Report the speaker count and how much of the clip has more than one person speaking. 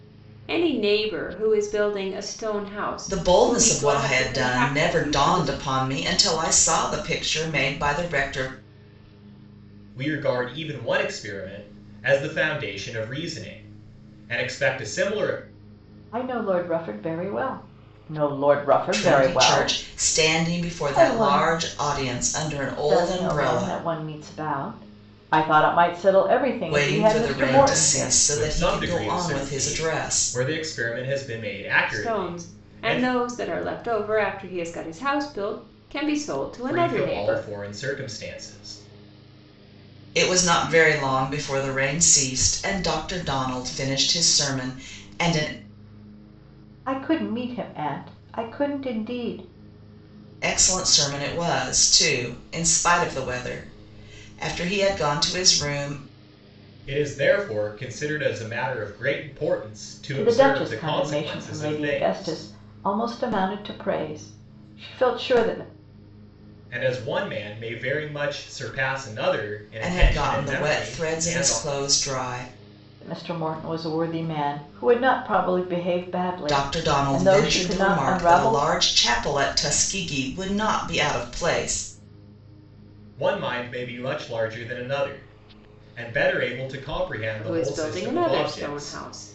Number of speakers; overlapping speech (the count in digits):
4, about 22%